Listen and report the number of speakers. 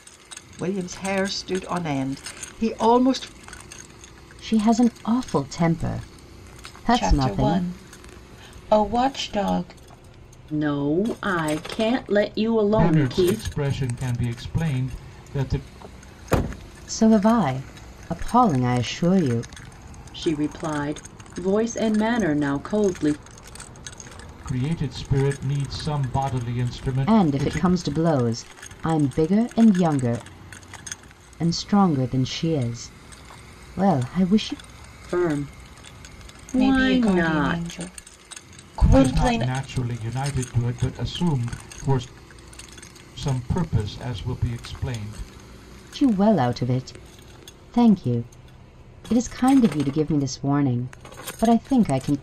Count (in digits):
5